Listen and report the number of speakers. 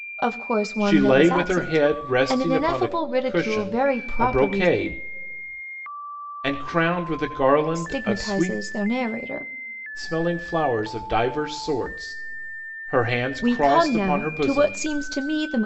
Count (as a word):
two